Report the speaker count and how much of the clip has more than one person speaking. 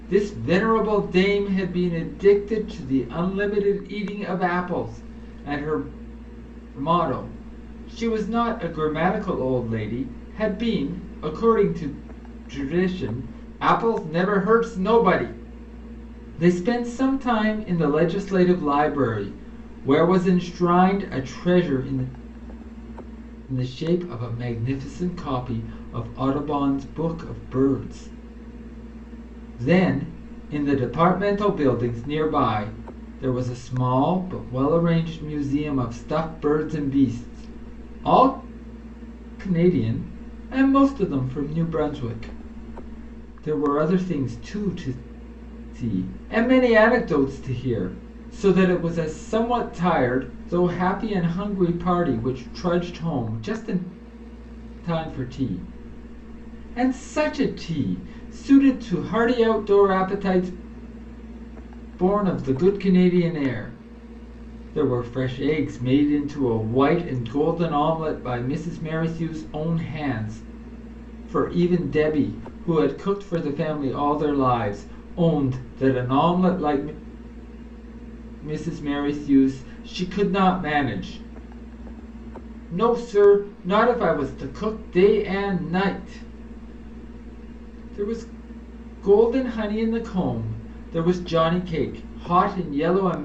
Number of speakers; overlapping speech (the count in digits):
1, no overlap